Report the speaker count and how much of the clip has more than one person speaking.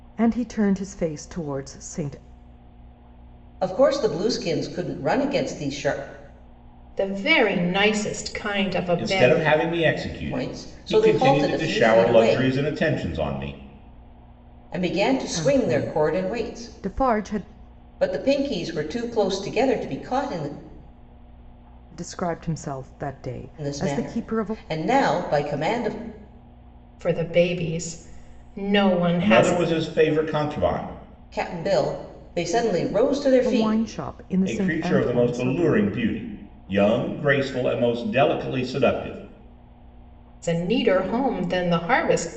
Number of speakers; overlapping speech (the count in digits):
4, about 18%